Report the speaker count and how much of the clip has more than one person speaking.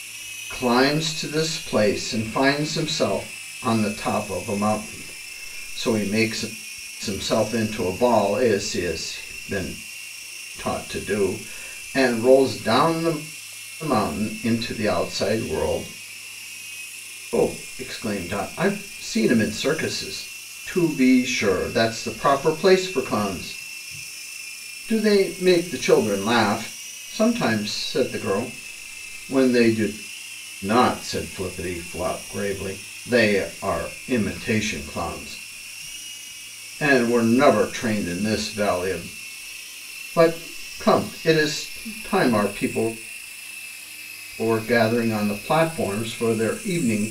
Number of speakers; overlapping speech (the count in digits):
1, no overlap